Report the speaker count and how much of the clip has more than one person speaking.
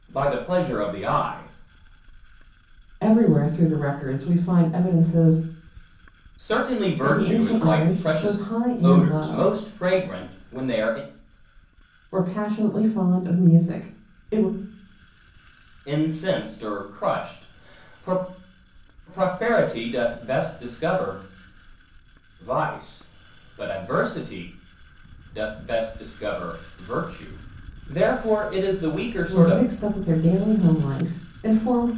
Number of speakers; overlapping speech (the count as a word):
two, about 8%